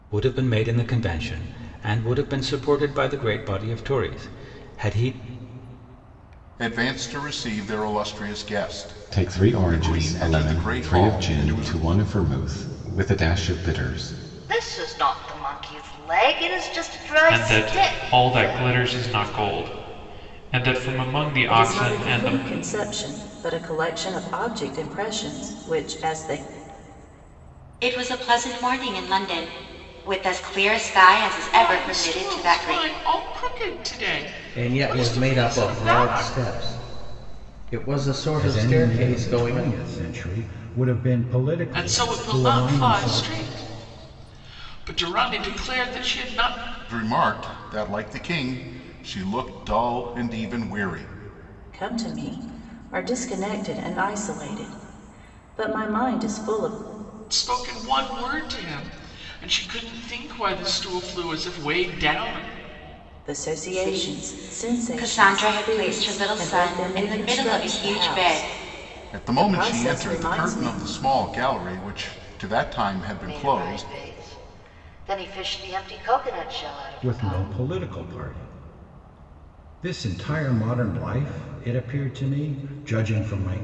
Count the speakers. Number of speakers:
ten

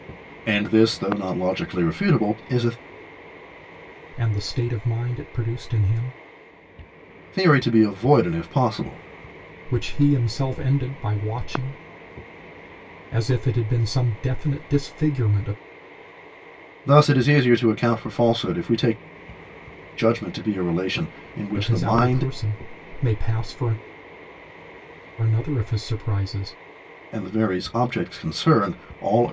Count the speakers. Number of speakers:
two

